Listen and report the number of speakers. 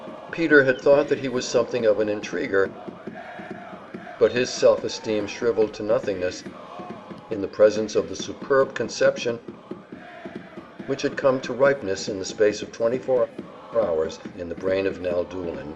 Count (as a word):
one